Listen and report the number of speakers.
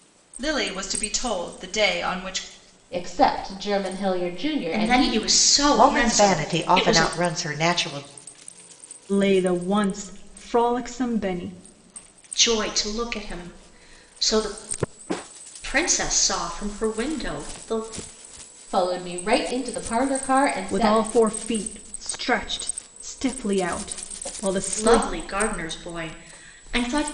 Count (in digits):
5